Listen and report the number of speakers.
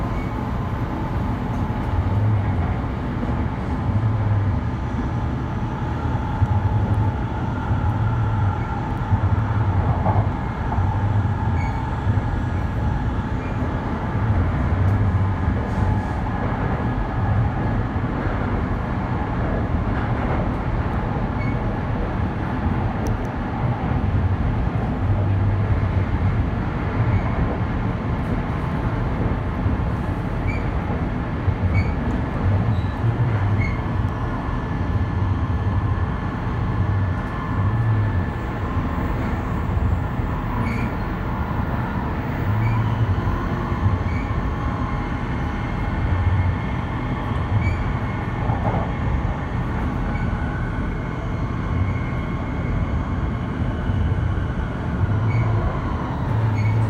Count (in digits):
0